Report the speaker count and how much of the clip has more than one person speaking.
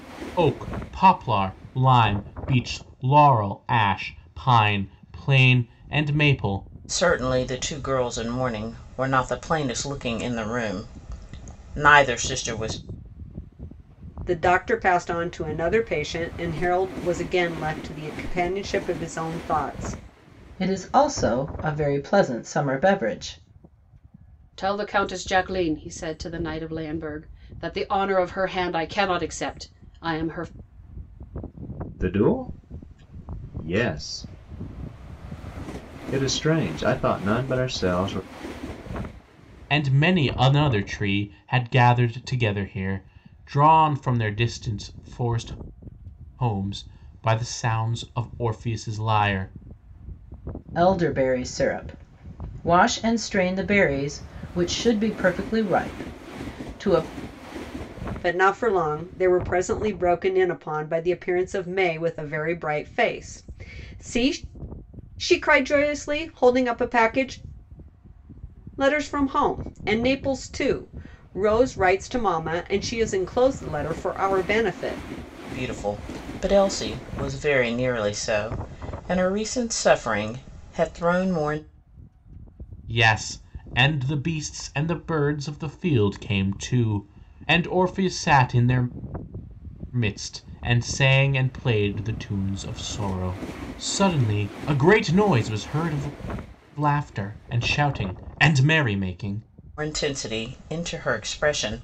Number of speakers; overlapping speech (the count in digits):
6, no overlap